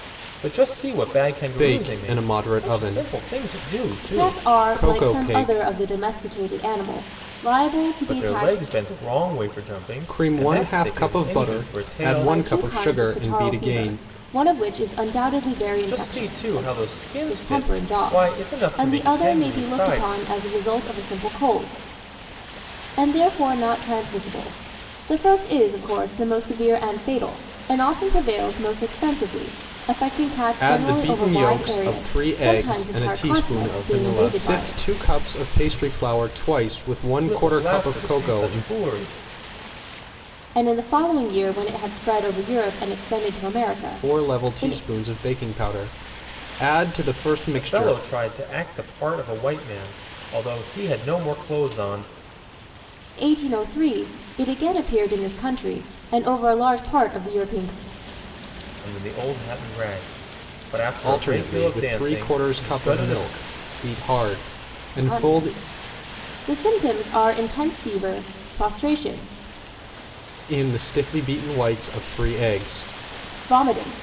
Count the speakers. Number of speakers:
three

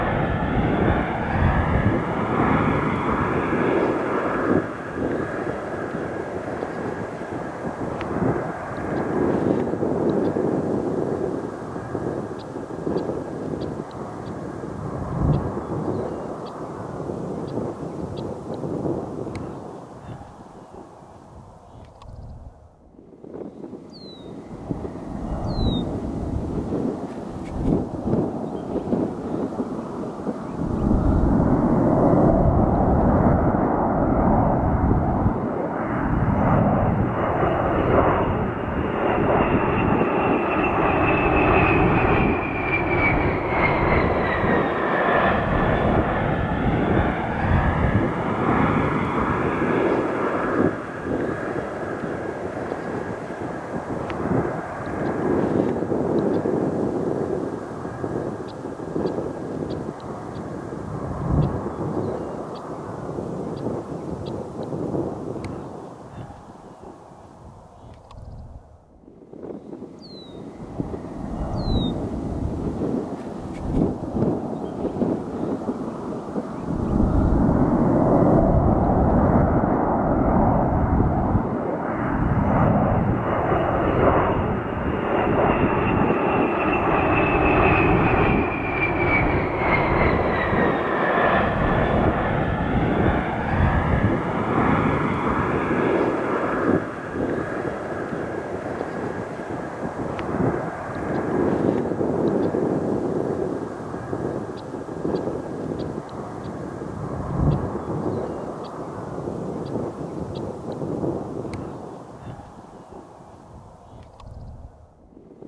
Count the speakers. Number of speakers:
zero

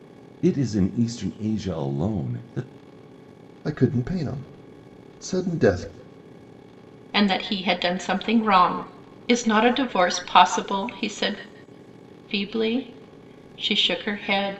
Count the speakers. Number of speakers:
three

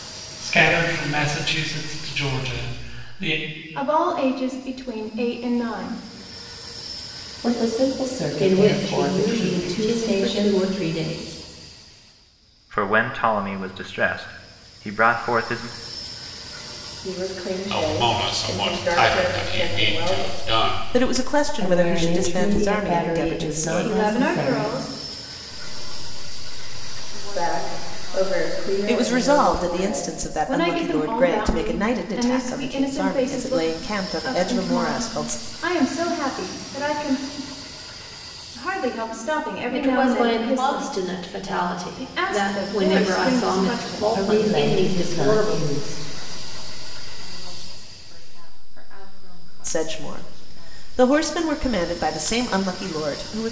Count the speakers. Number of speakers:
nine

